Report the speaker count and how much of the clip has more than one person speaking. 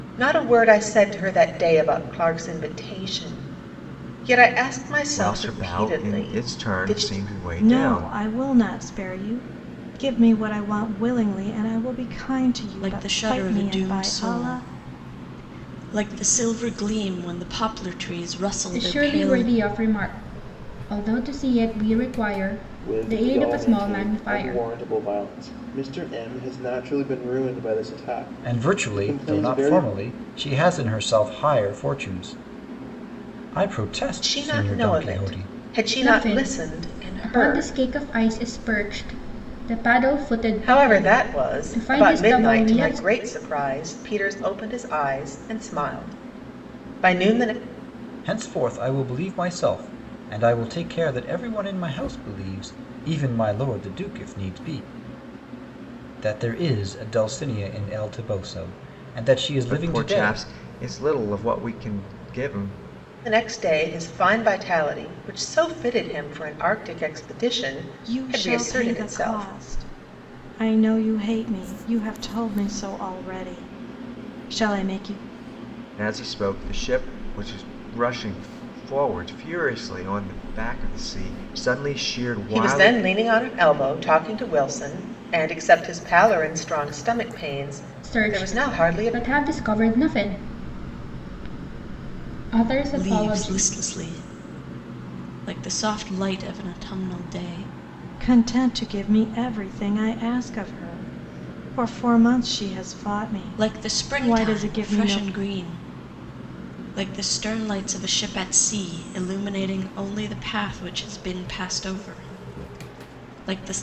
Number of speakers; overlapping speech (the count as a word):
seven, about 18%